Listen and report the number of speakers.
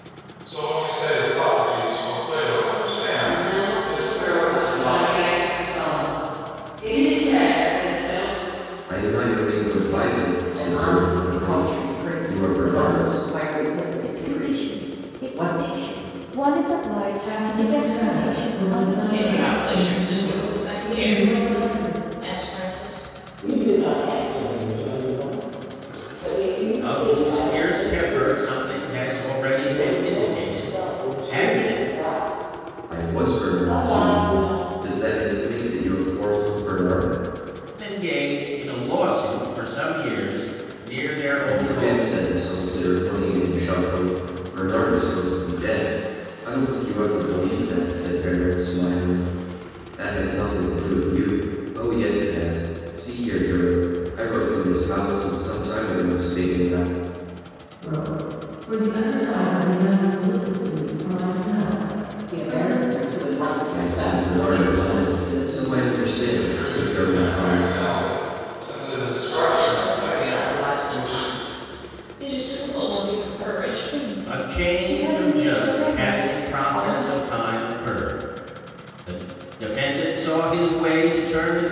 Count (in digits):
9